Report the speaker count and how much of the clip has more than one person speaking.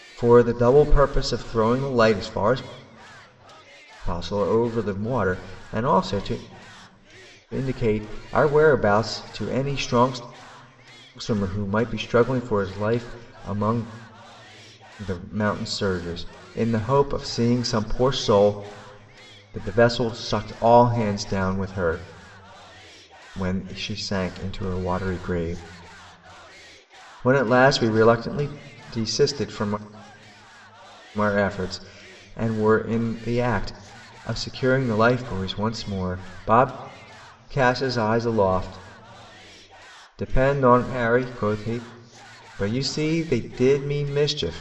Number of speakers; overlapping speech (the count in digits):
1, no overlap